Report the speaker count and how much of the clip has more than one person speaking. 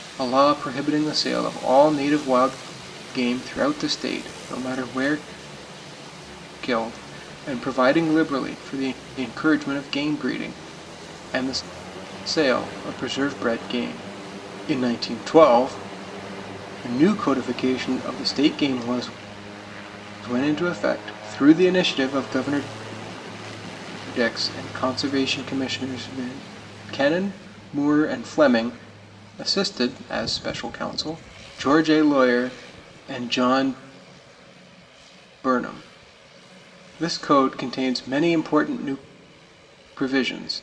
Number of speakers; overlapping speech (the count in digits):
1, no overlap